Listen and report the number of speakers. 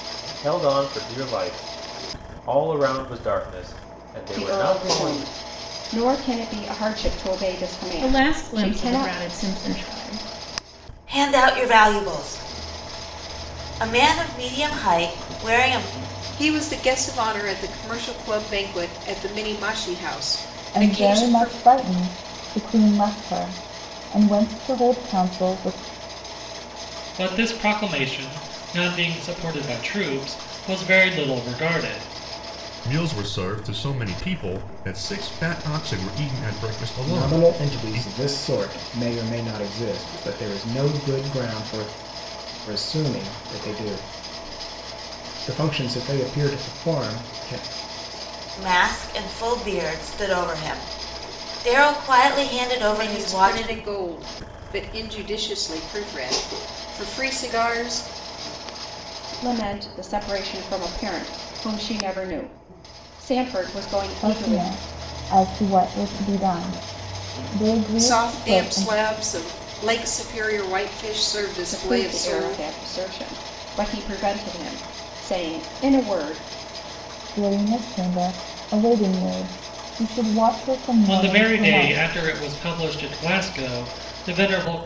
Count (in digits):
9